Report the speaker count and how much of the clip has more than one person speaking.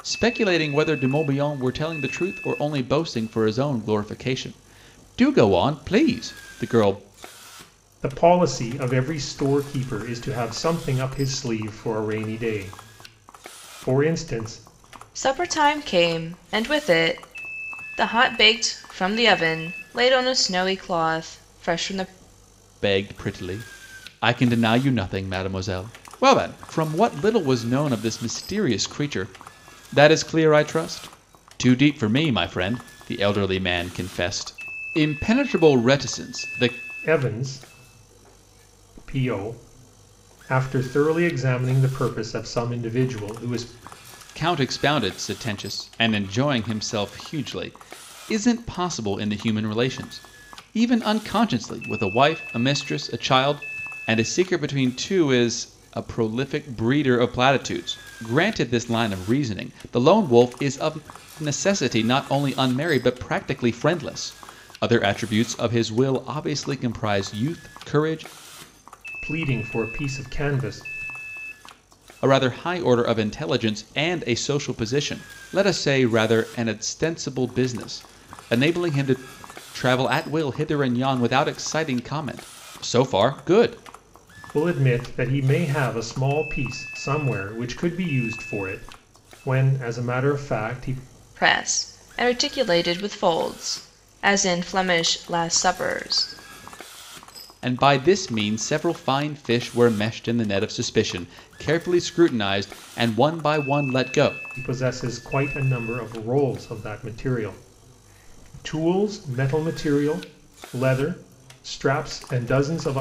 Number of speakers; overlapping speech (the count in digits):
3, no overlap